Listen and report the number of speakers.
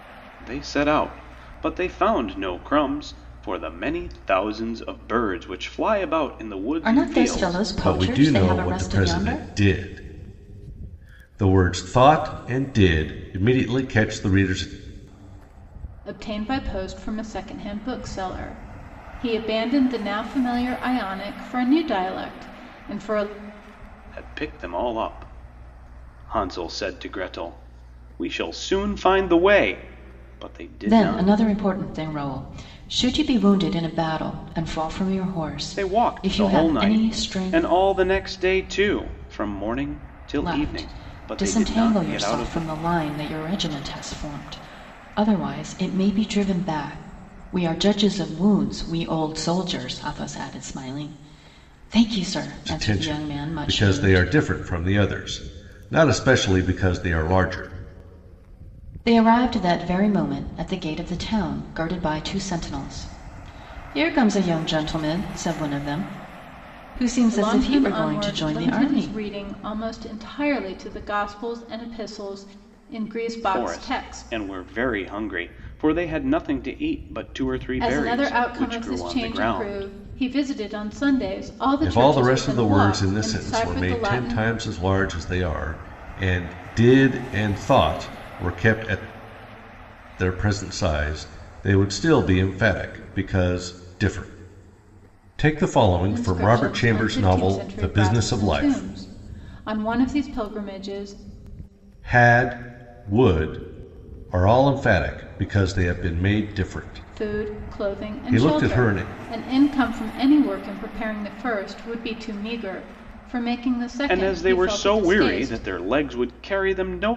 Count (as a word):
four